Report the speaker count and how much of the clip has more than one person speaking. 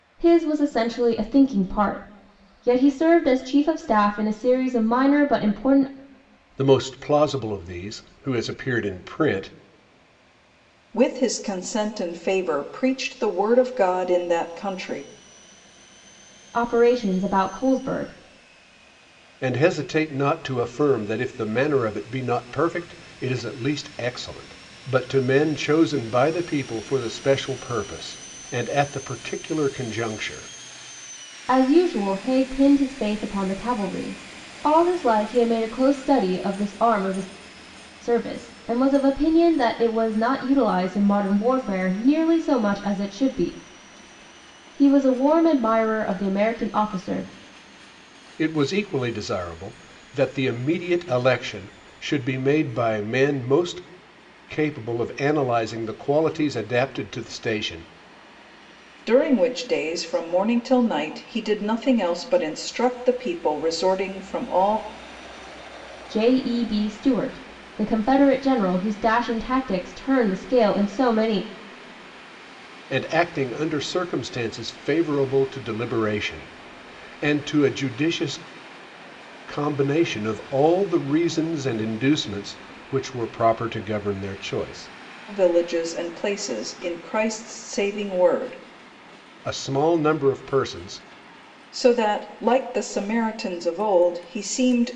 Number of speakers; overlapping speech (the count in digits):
3, no overlap